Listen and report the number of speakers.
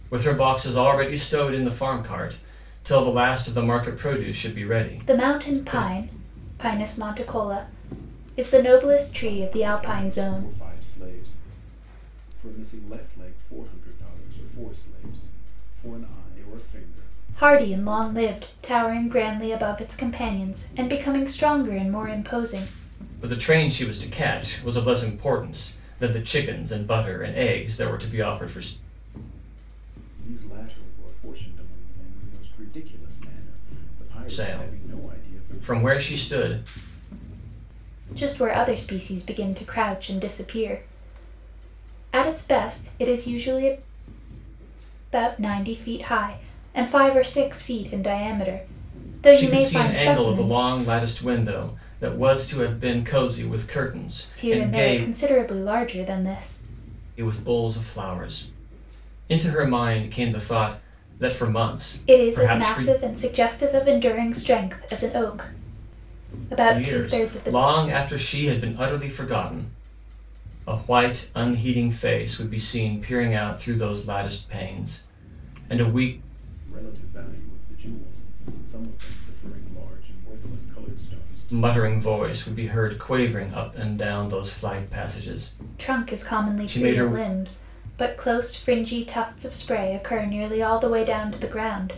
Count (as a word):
three